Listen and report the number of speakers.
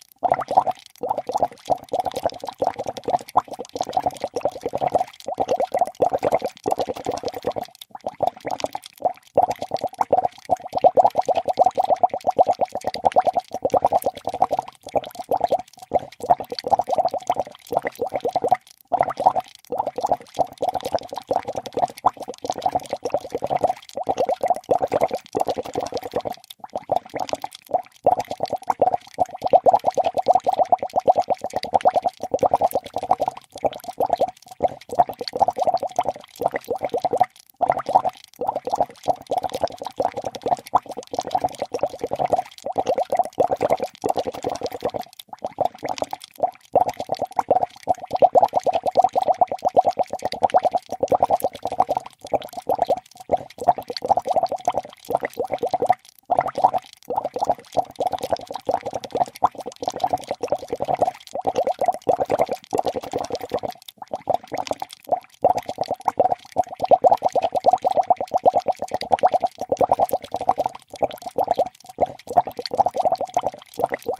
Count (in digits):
0